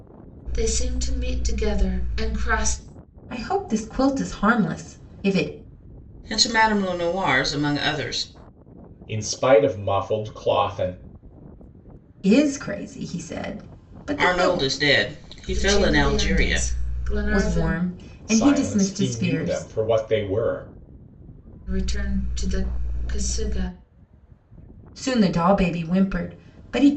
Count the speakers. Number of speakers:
4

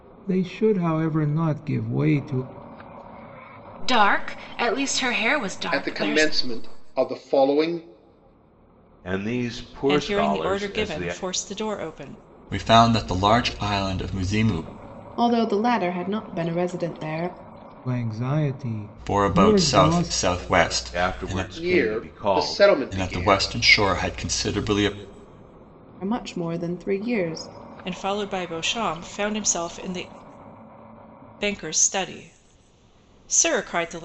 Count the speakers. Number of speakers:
7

